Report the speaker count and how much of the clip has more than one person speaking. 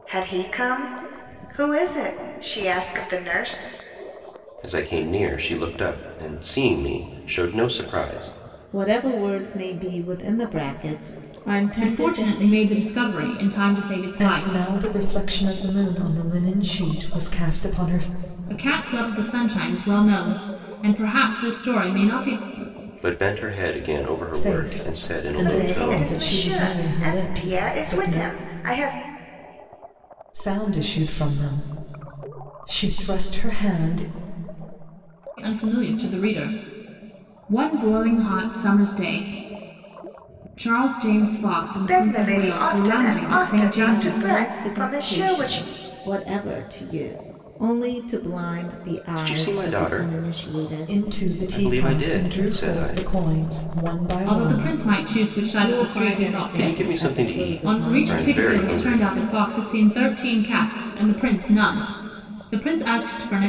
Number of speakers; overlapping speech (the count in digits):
5, about 26%